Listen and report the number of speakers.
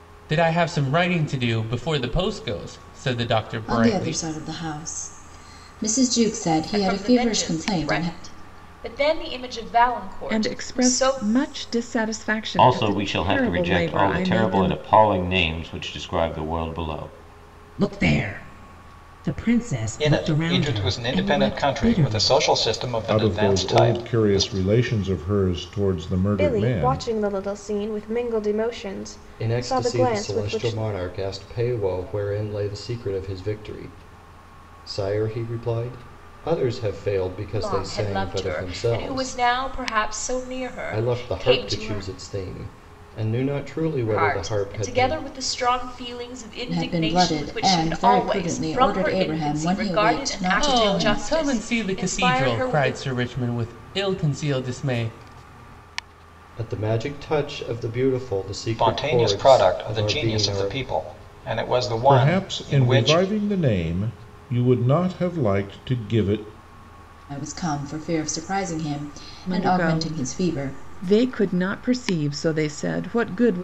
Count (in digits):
10